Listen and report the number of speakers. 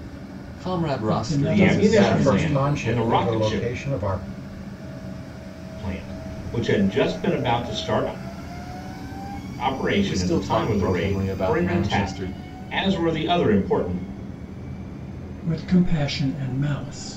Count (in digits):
4